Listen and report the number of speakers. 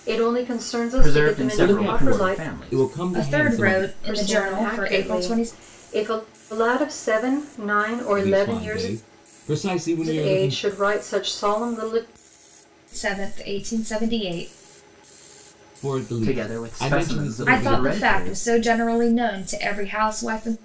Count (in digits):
4